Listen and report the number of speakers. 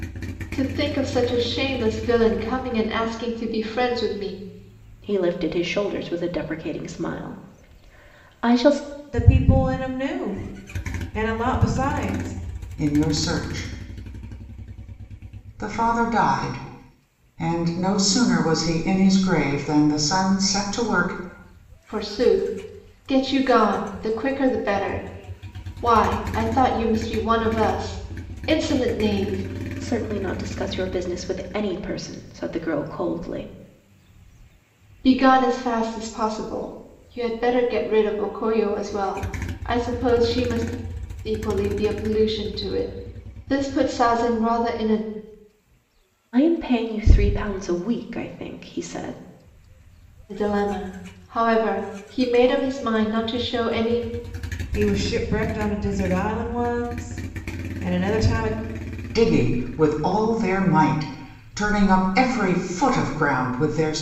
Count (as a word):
four